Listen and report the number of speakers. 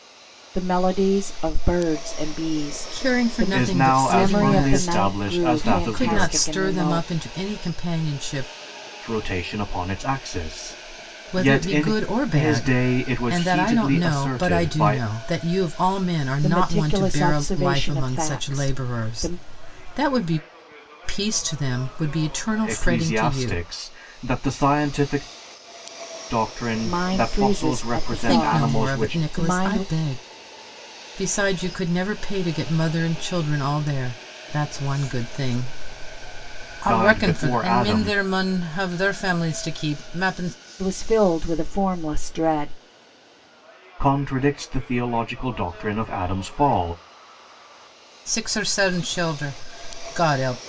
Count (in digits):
3